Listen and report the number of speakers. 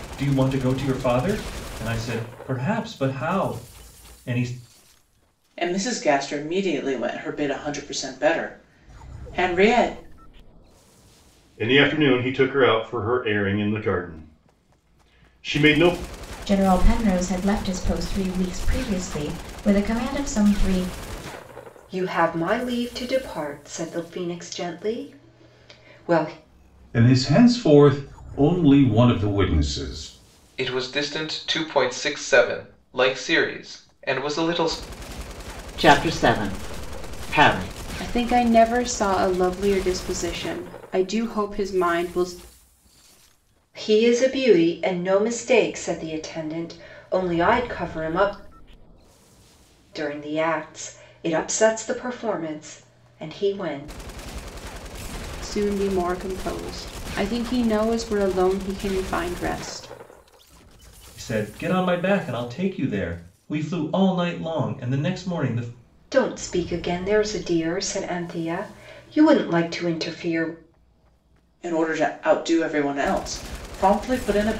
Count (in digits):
9